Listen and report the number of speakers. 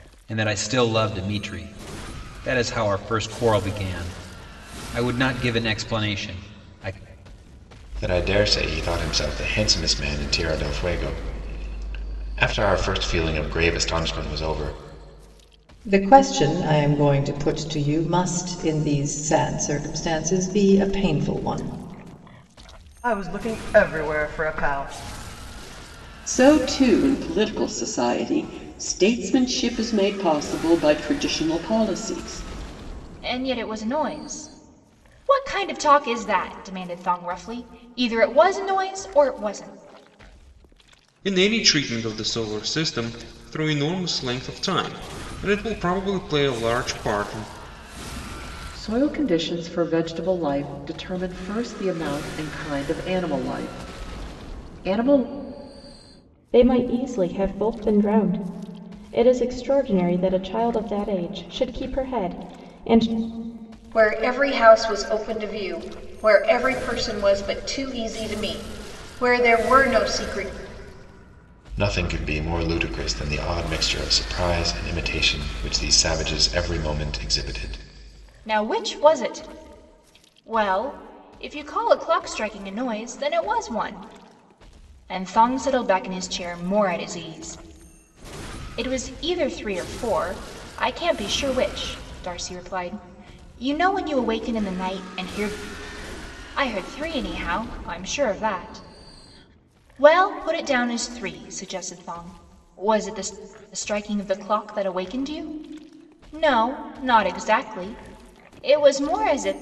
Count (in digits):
10